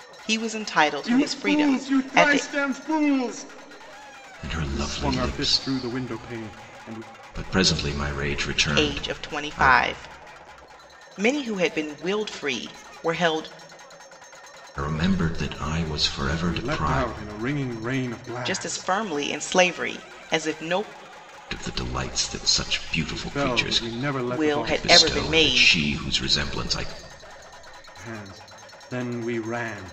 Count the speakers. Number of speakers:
3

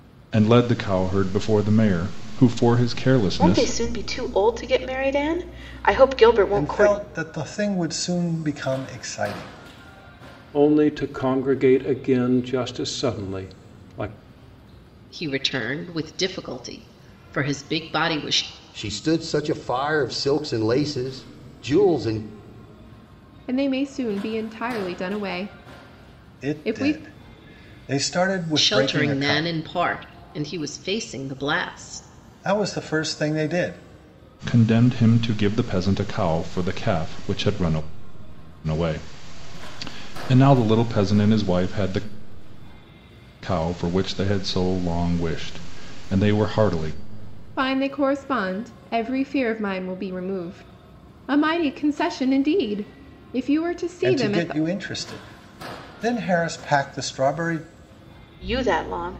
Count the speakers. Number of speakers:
7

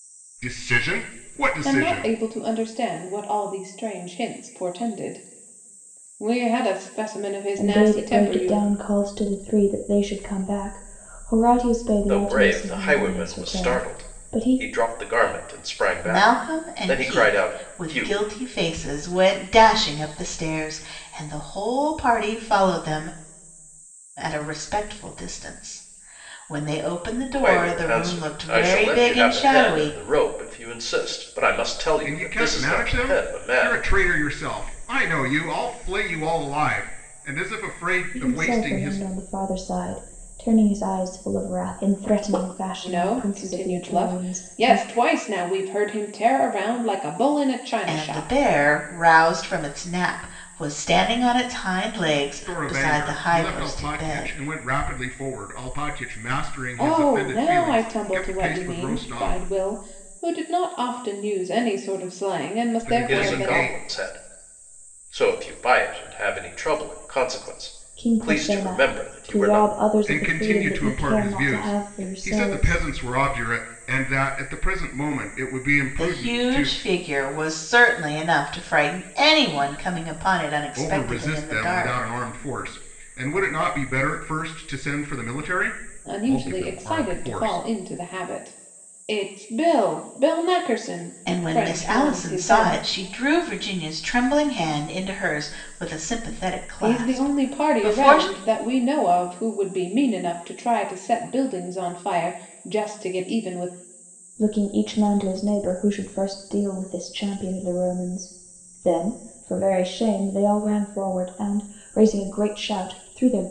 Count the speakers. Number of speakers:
5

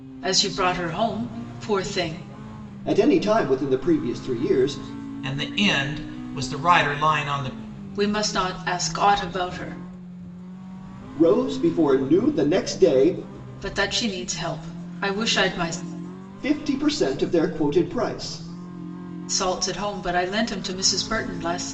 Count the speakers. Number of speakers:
3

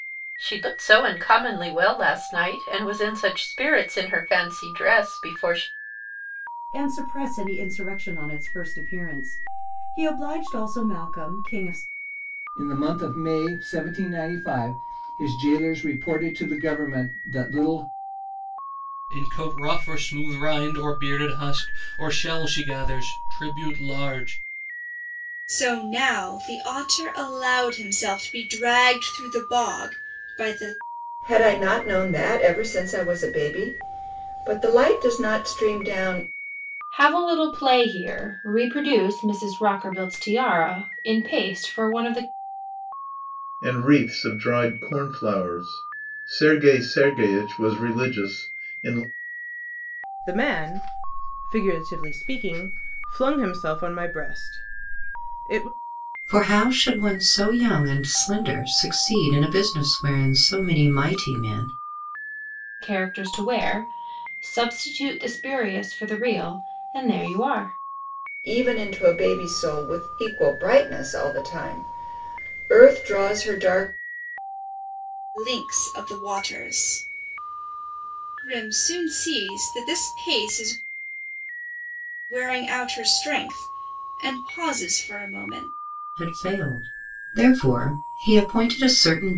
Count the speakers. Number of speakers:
10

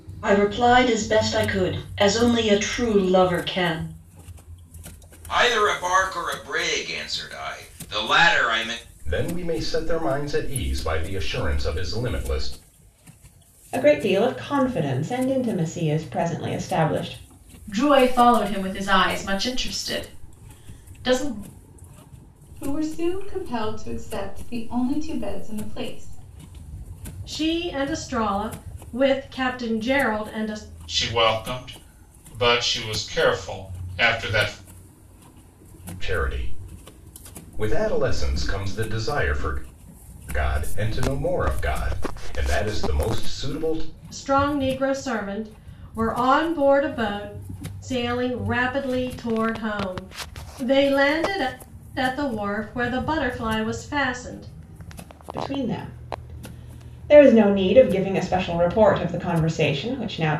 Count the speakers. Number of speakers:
8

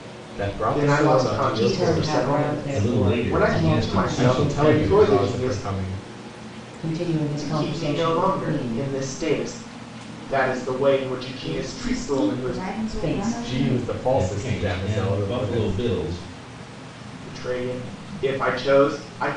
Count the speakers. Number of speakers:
5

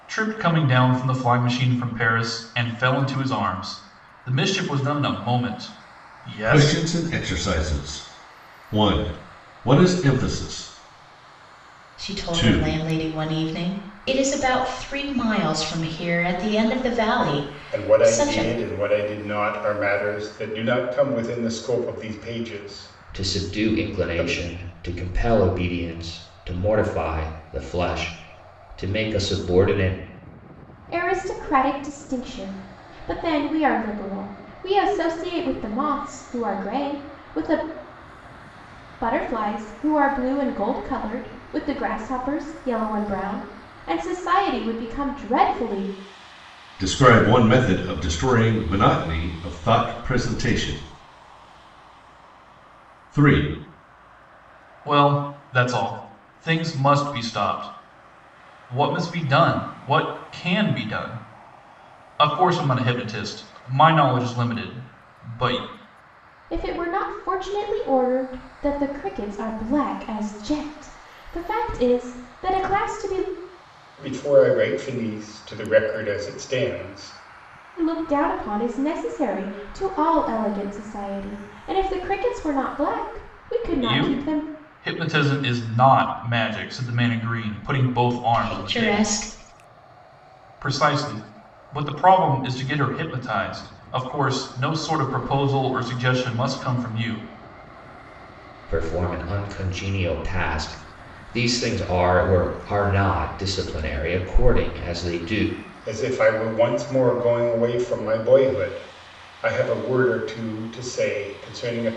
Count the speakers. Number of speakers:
6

